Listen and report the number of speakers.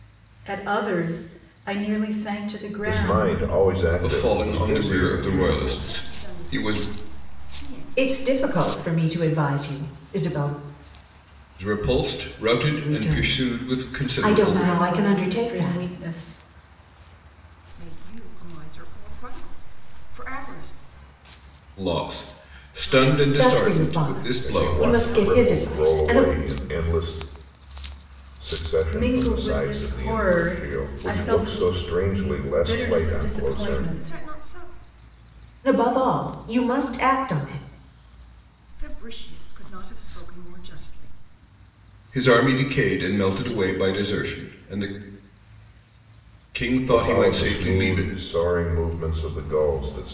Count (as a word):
five